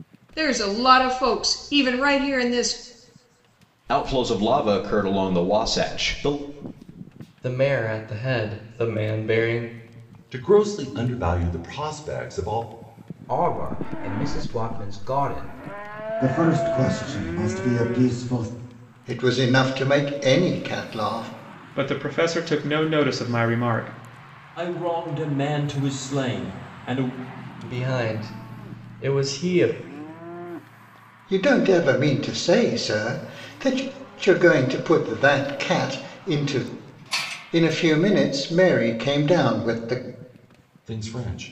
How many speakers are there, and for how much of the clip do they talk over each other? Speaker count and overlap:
nine, no overlap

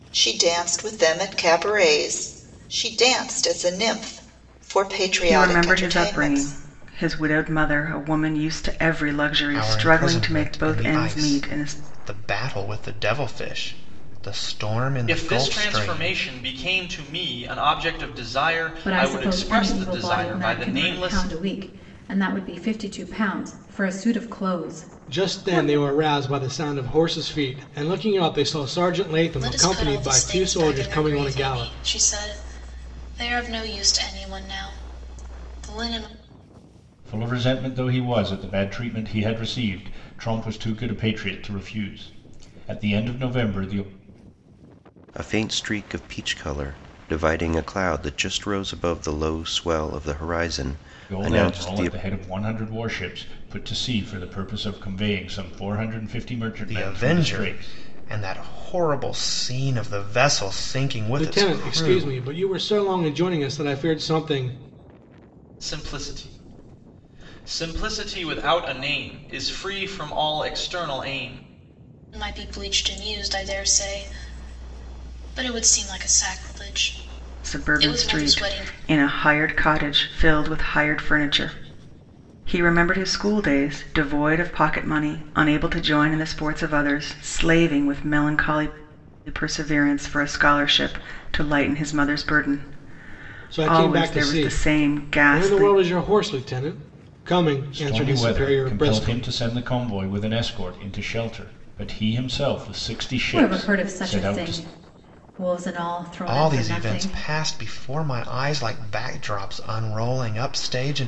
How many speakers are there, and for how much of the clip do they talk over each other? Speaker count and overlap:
nine, about 19%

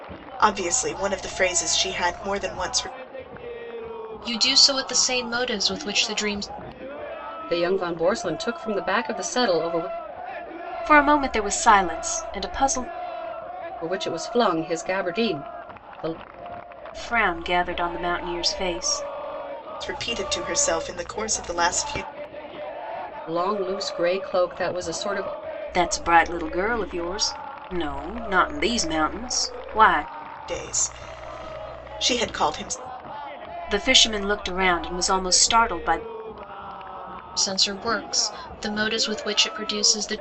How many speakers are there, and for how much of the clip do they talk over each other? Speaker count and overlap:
four, no overlap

